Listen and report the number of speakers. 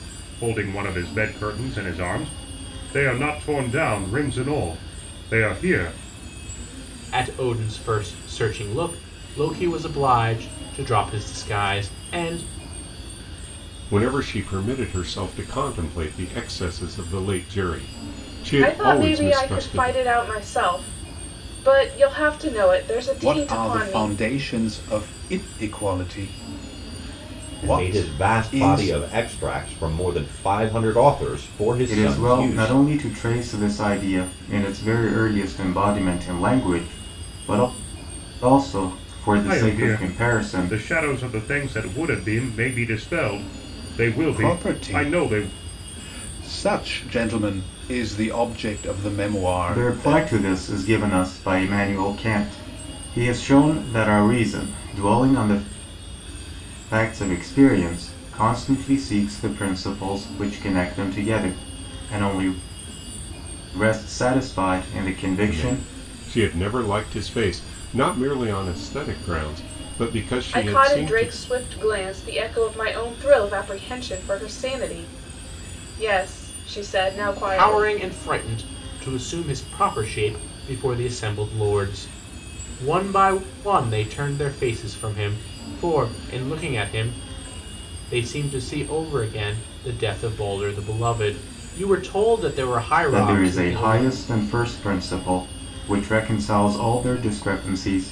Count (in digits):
7